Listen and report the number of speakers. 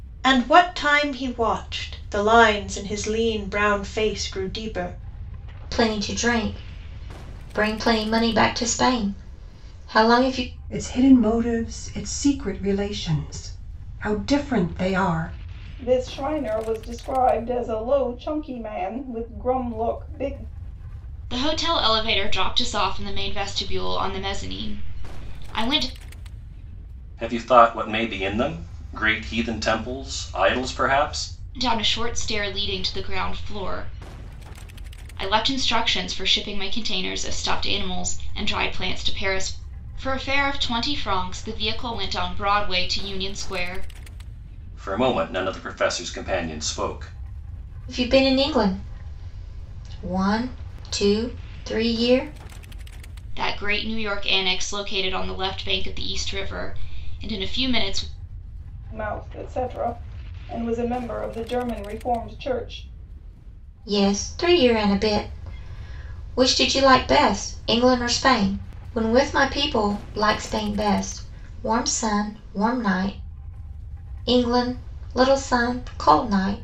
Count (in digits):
6